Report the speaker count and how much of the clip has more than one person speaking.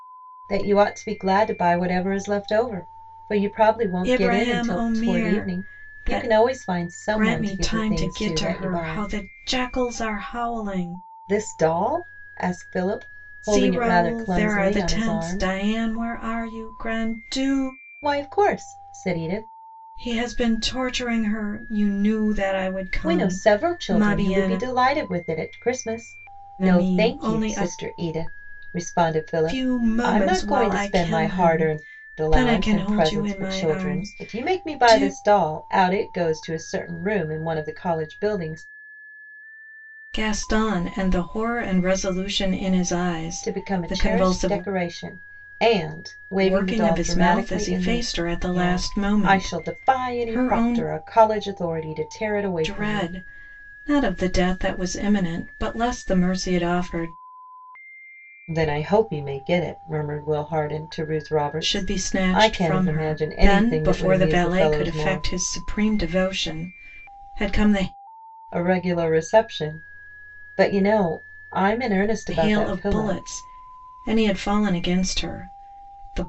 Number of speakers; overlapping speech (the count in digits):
2, about 32%